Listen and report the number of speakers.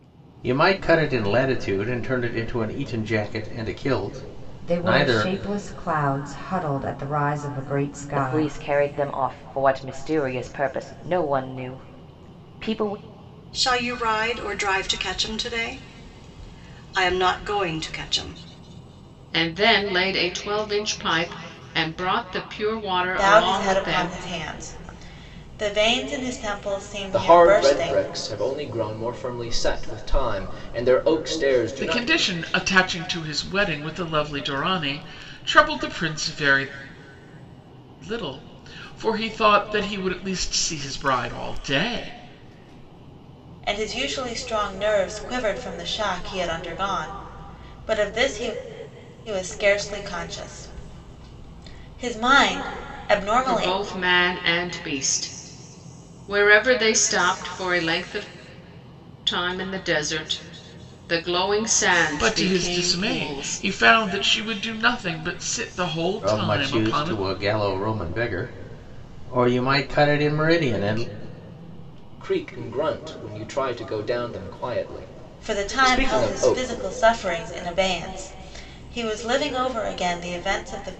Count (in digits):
8